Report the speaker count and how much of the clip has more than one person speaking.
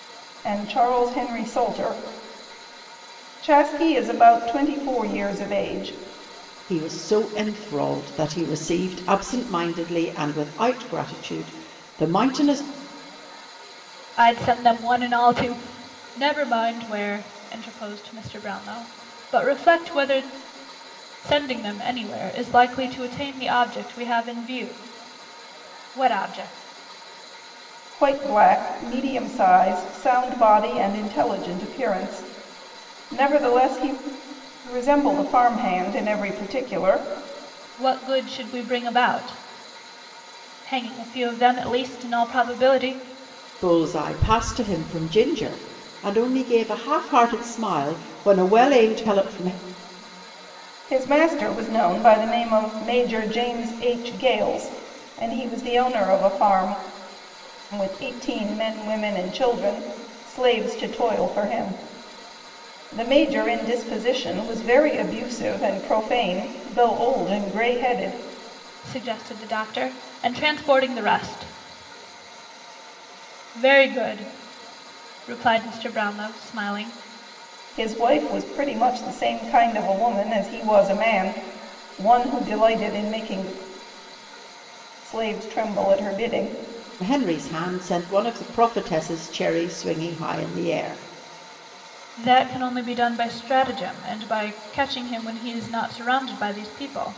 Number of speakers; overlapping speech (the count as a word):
three, no overlap